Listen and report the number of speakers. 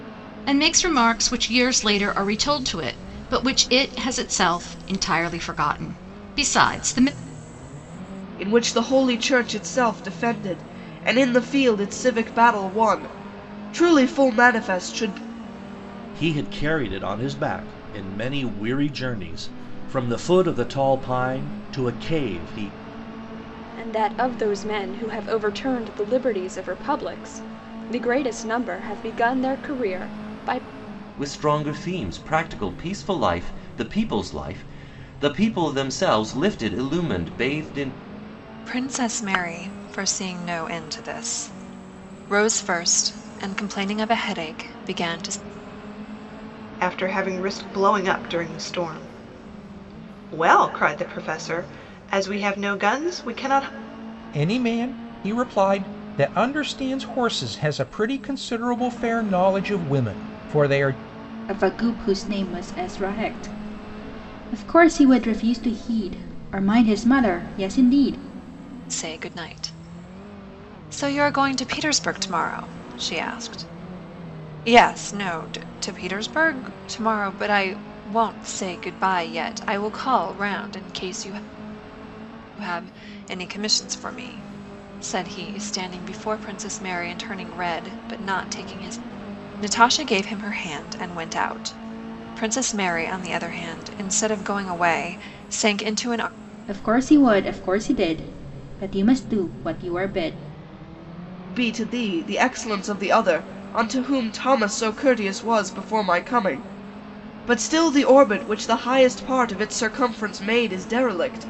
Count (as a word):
nine